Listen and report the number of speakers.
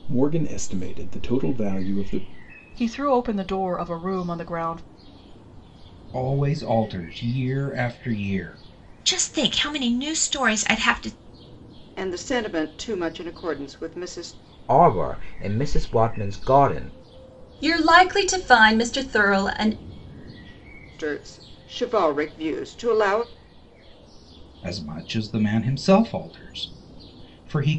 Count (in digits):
7